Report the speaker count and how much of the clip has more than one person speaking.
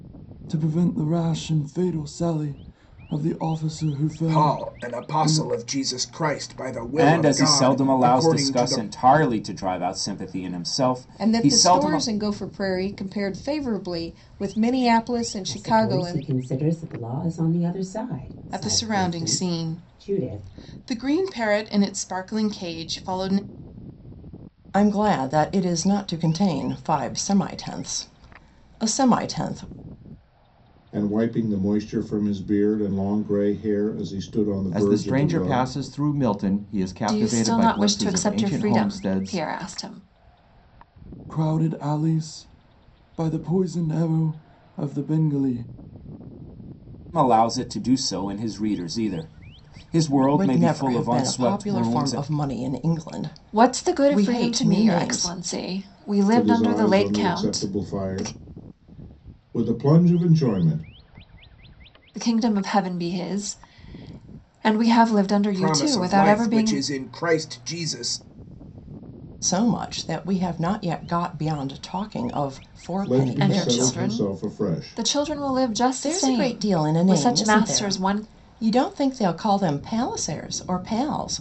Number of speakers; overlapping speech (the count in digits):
10, about 27%